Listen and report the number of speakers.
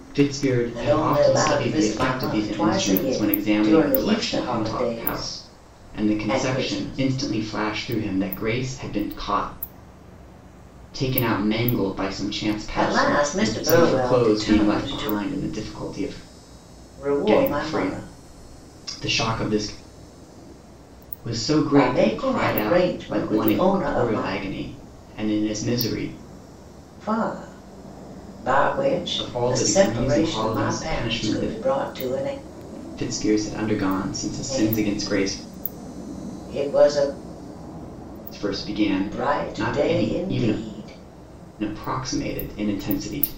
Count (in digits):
2